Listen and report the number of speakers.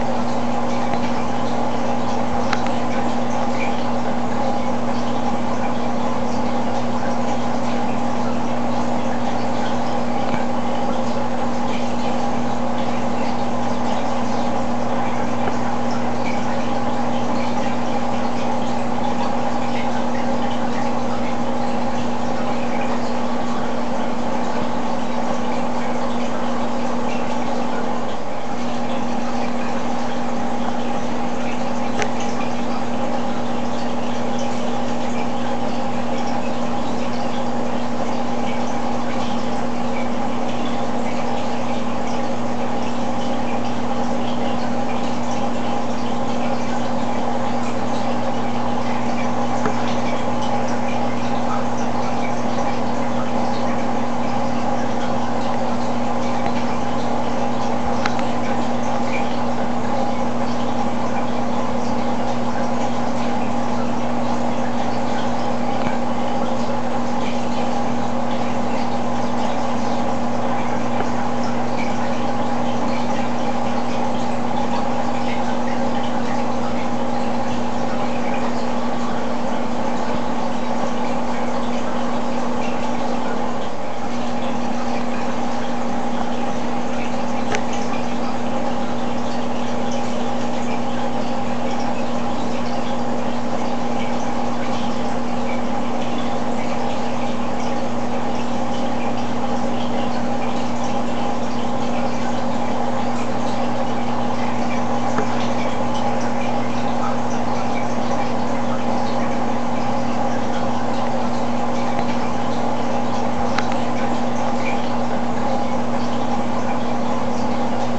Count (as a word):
zero